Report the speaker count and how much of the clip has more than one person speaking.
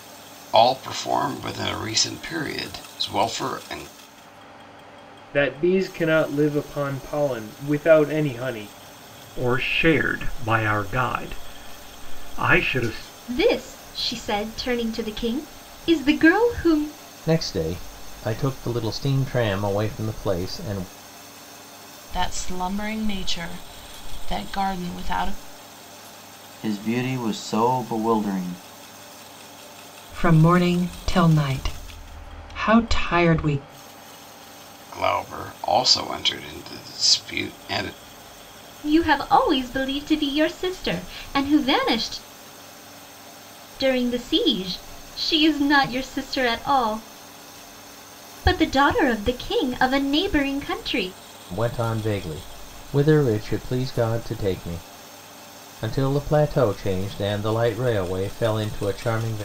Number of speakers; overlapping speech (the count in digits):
8, no overlap